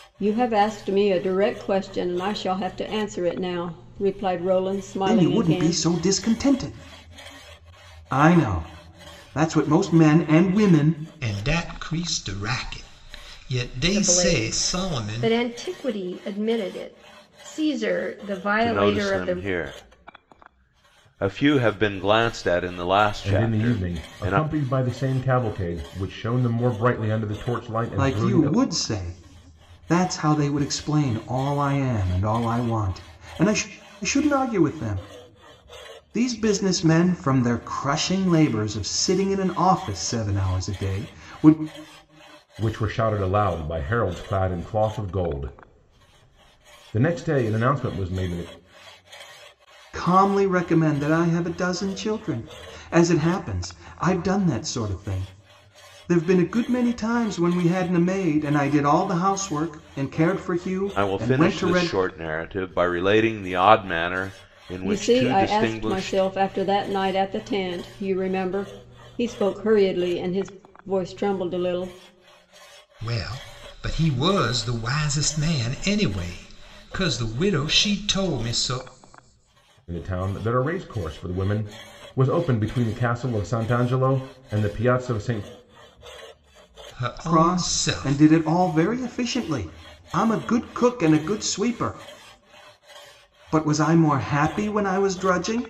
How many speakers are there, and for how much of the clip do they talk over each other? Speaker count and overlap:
6, about 9%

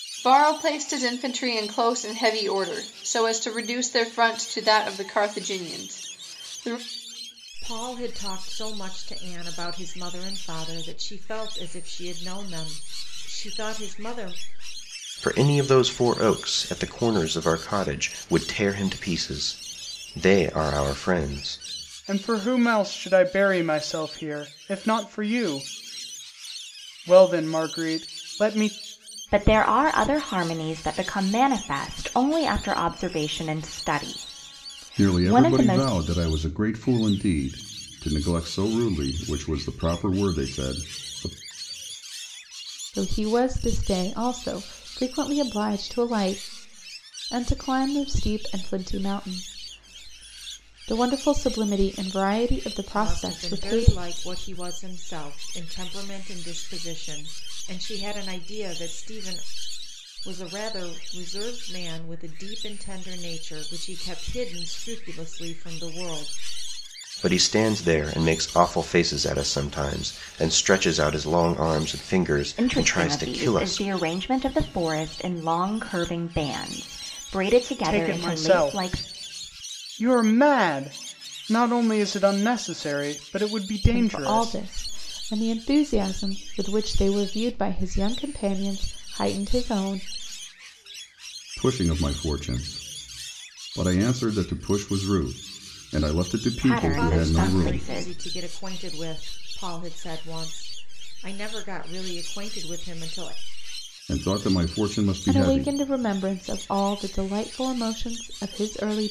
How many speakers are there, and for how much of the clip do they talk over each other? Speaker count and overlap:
7, about 7%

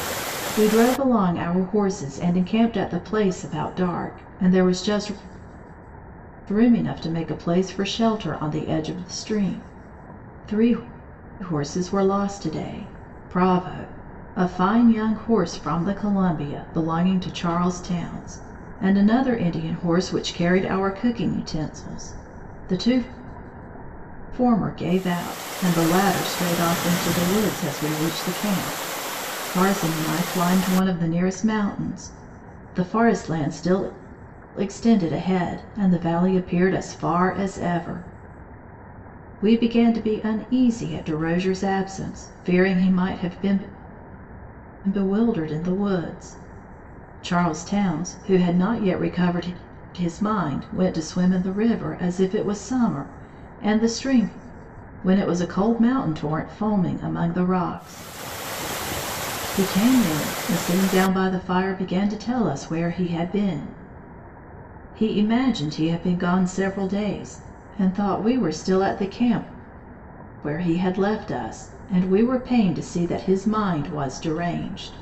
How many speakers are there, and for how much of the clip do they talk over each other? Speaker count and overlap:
1, no overlap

